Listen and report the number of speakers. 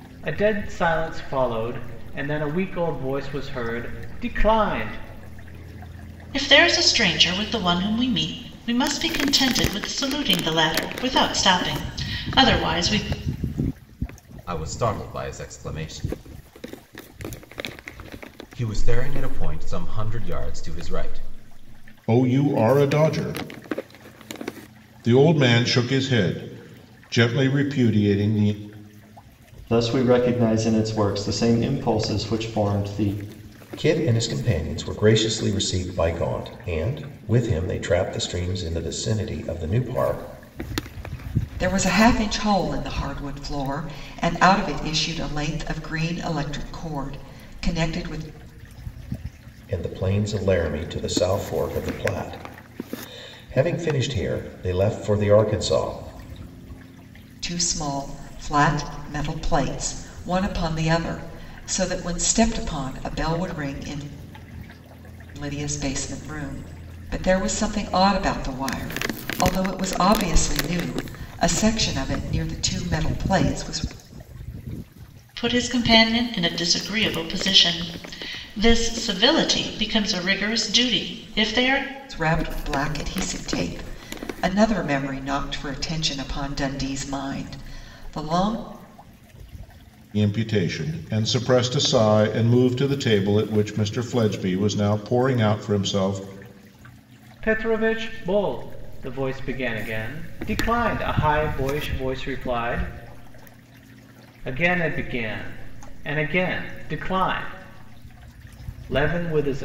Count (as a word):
seven